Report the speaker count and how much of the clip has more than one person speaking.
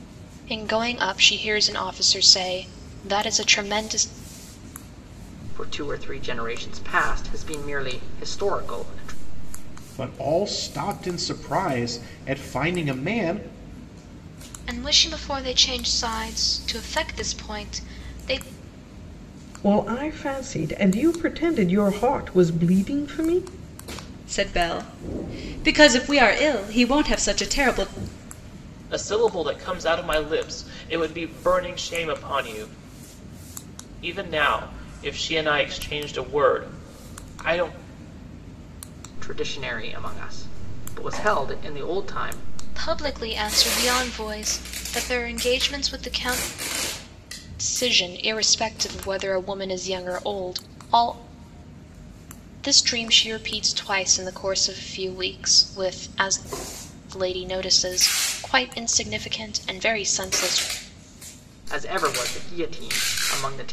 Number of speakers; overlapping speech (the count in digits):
7, no overlap